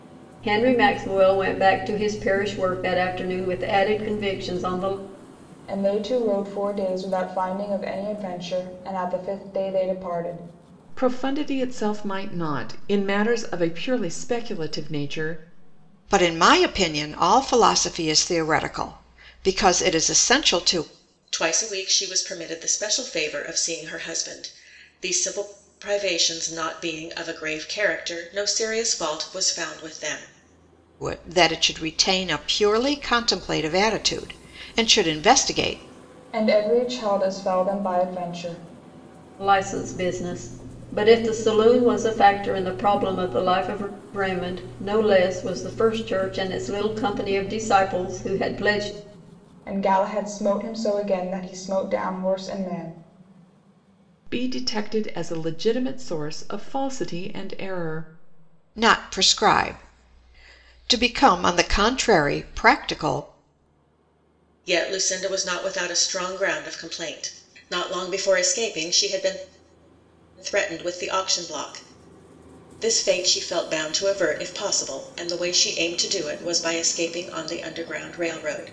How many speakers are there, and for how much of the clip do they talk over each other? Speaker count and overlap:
5, no overlap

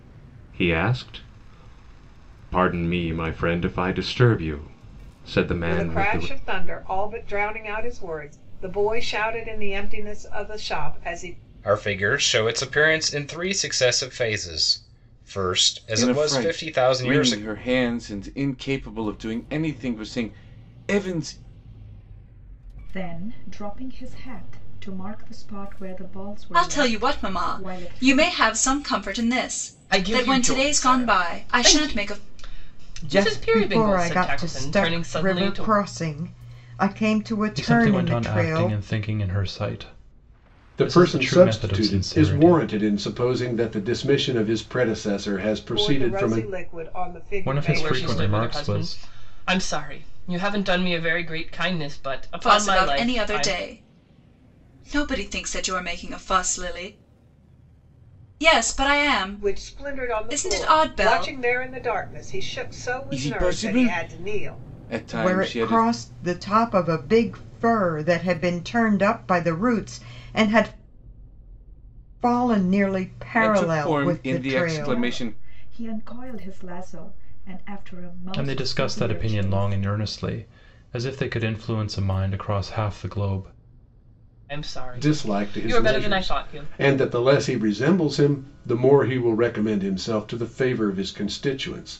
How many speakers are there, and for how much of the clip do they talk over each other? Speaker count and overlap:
10, about 27%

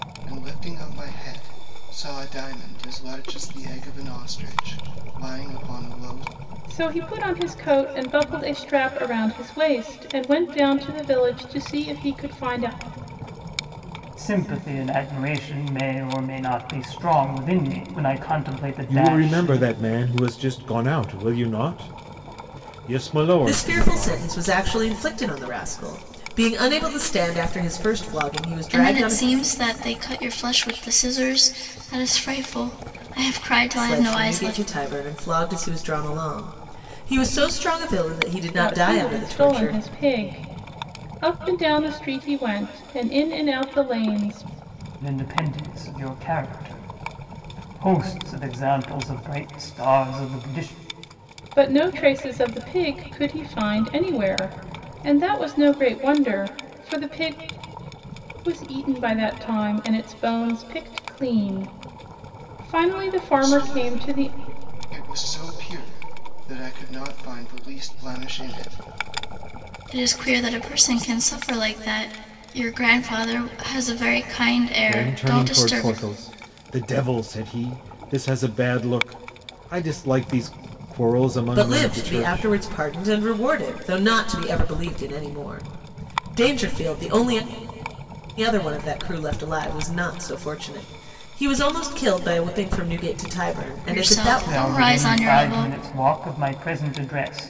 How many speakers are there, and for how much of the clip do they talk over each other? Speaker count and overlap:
6, about 10%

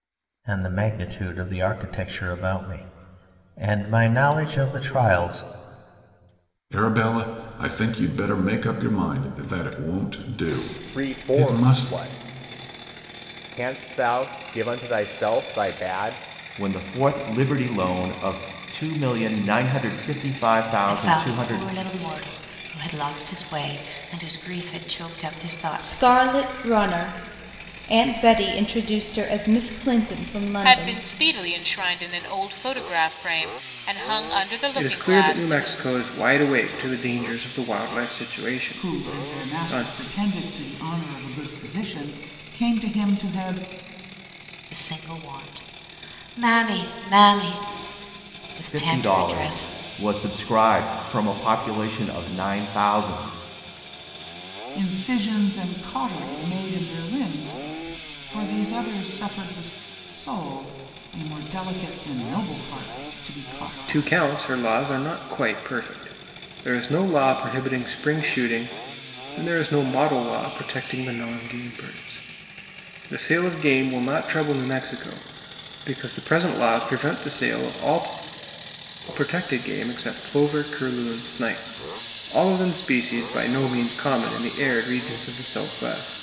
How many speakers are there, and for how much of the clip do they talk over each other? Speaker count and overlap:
9, about 8%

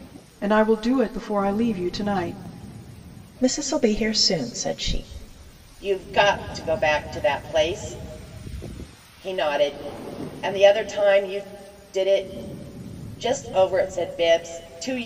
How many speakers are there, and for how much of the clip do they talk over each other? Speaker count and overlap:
3, no overlap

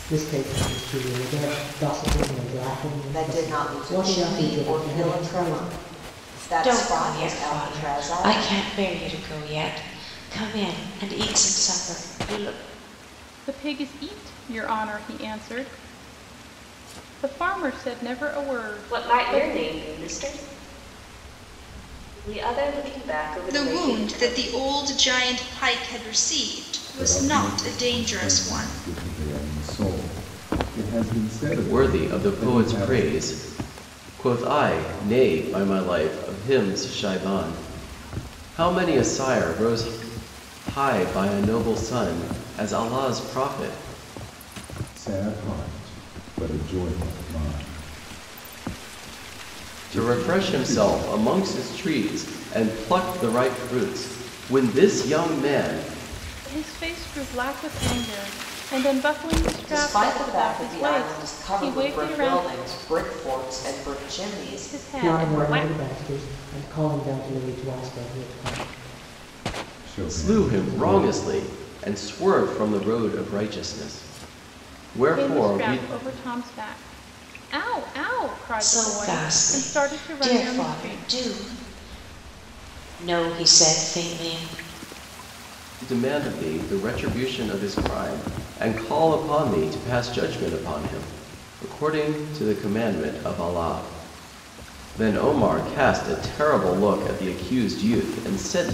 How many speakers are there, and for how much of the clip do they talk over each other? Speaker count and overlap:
8, about 20%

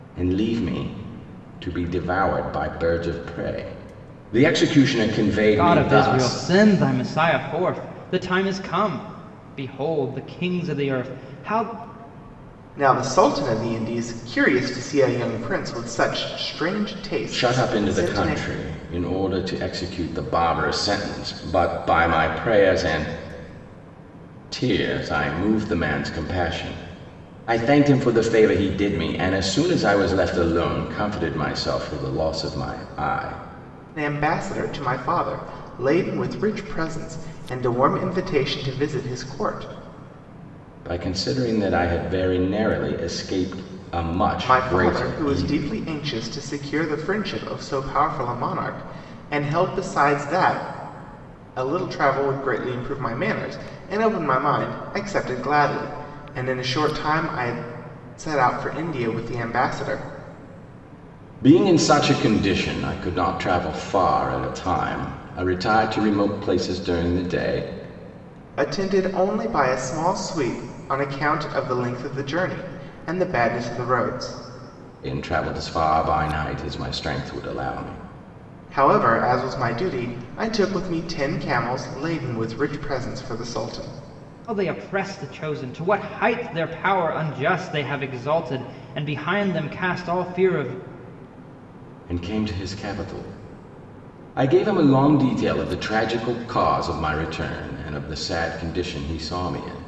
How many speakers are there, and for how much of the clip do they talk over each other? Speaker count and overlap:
3, about 3%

